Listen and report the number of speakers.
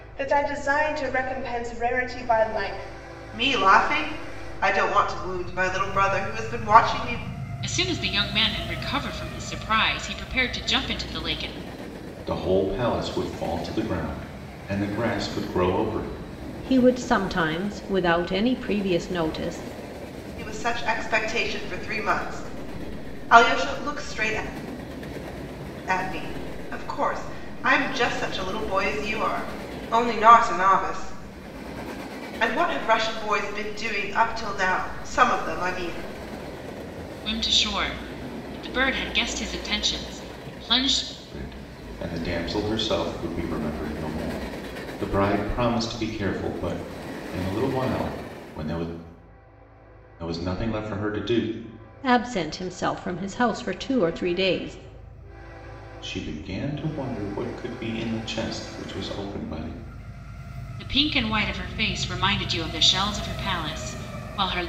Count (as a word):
five